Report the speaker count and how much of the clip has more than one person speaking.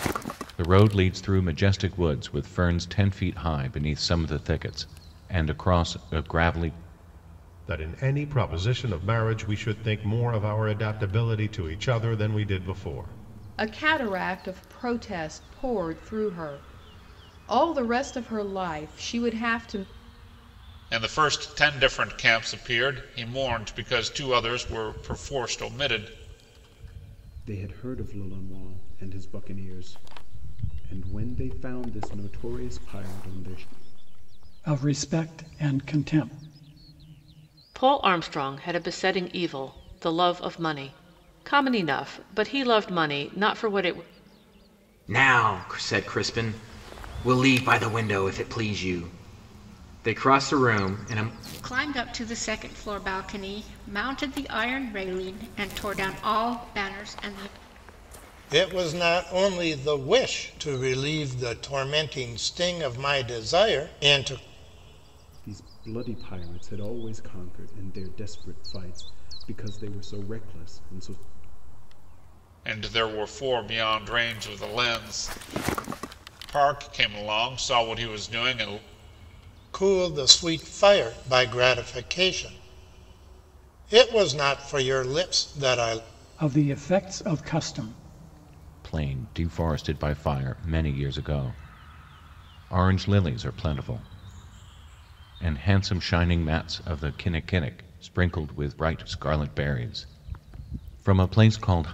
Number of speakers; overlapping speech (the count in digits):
10, no overlap